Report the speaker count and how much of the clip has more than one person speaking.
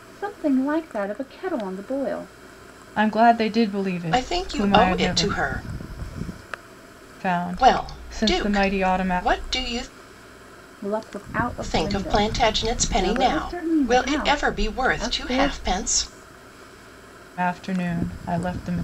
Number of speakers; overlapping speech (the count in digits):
3, about 35%